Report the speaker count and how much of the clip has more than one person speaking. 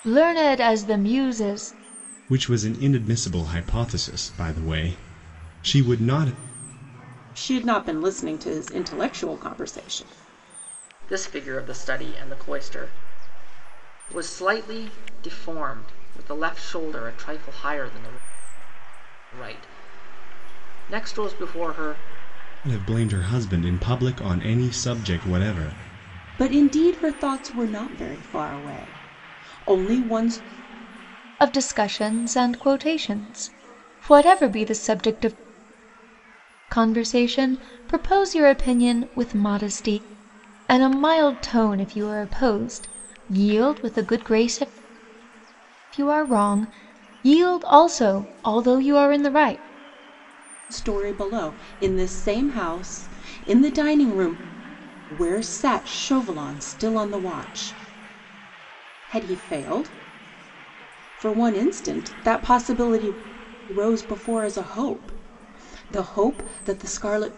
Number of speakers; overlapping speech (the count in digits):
4, no overlap